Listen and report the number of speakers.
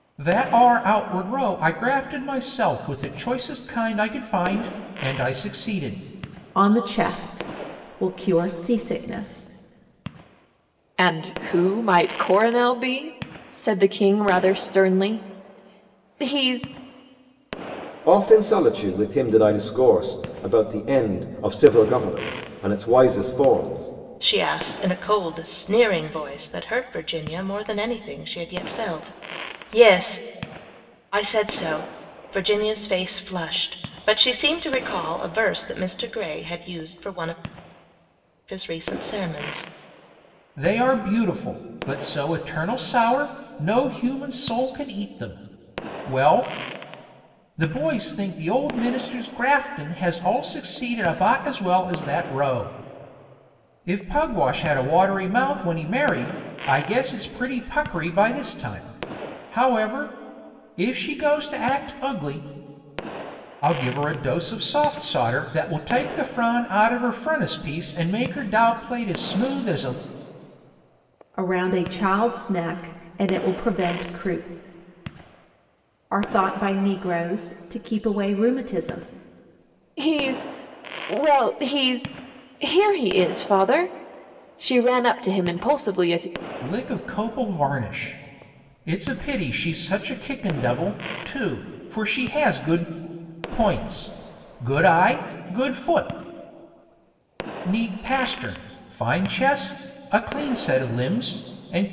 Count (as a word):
five